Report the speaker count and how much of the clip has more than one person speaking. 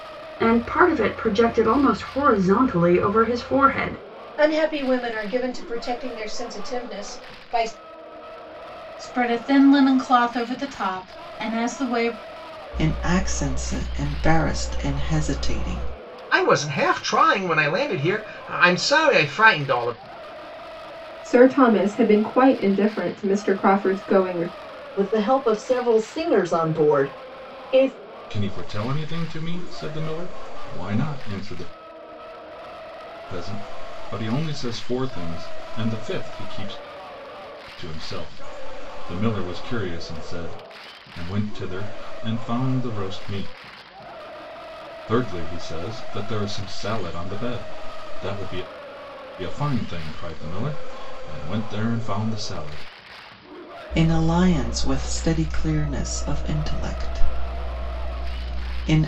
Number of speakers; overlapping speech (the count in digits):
8, no overlap